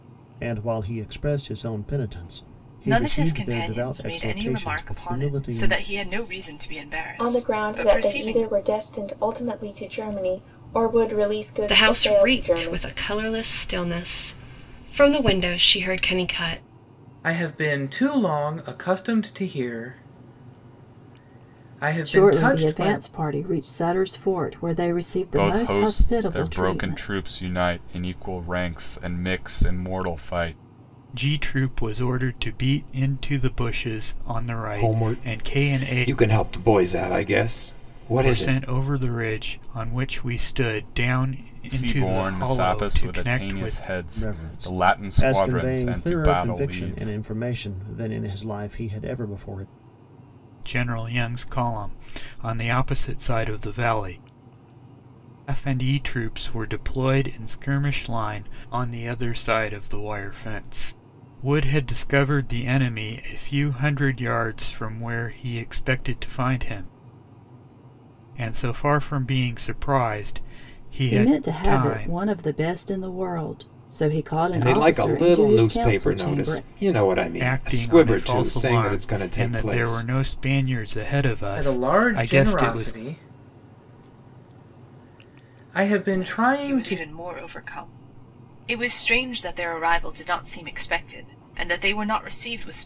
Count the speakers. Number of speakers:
9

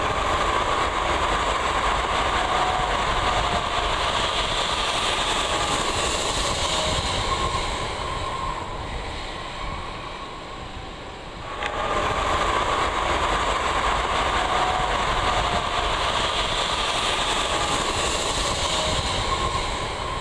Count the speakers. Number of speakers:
0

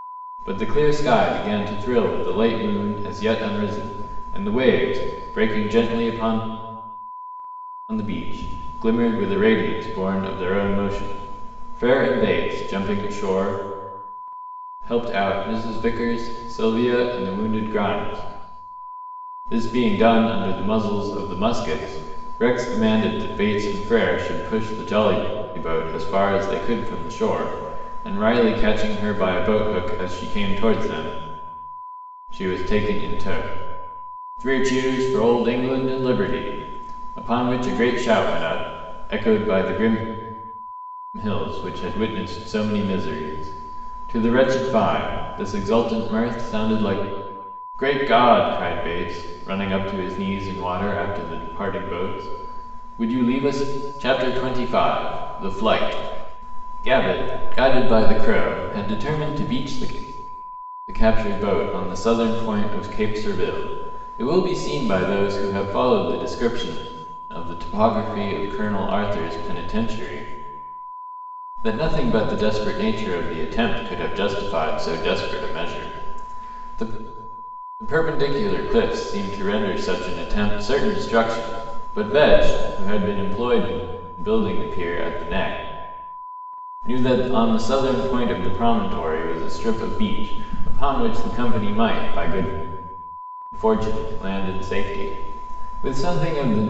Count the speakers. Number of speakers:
1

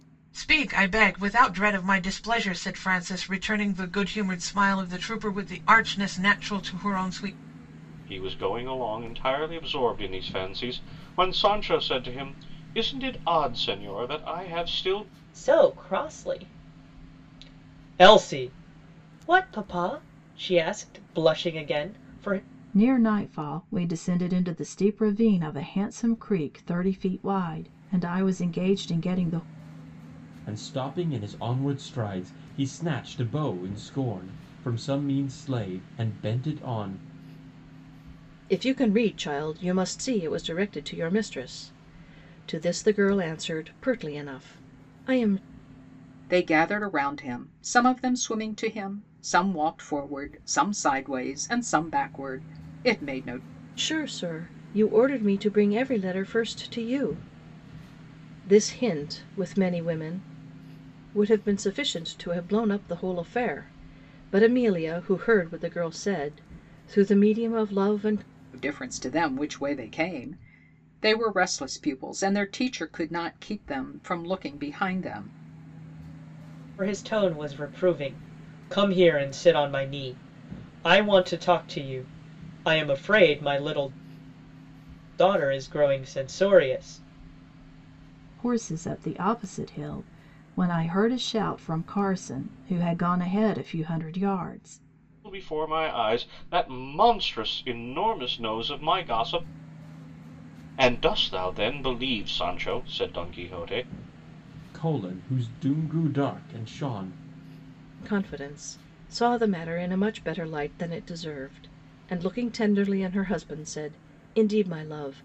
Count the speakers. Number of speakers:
7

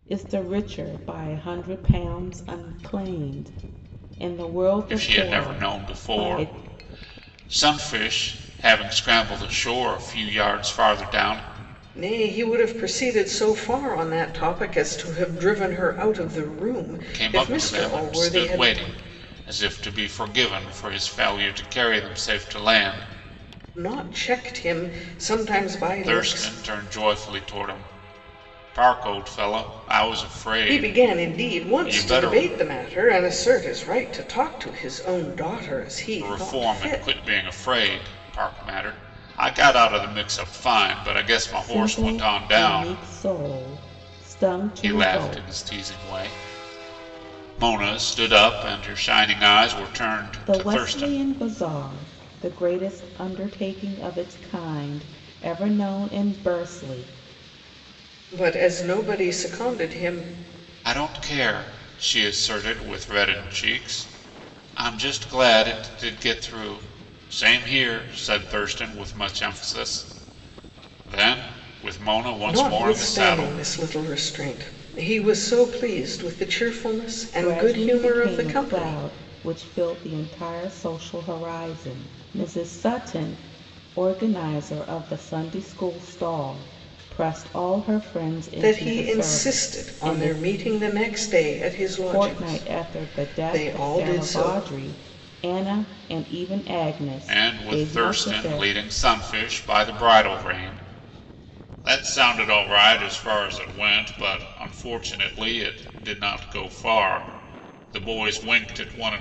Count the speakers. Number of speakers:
3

